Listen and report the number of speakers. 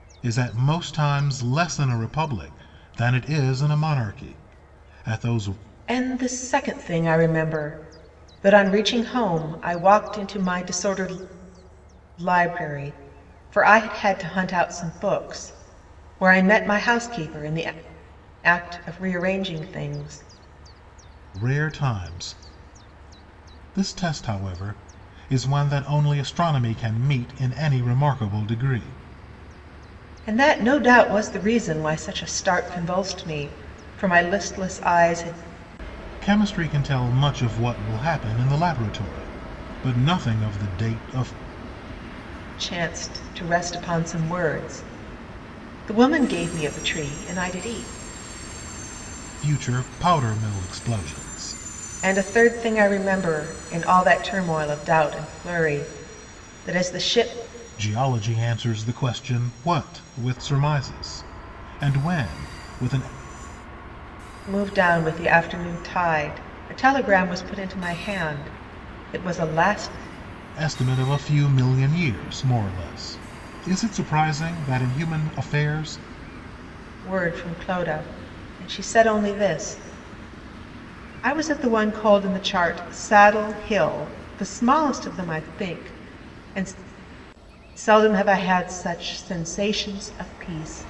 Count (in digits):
2